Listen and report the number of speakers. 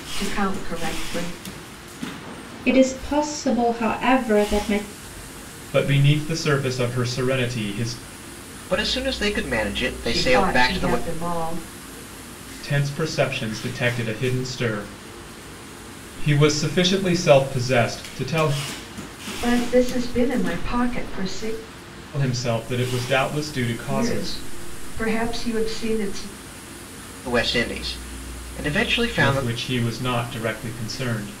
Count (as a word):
four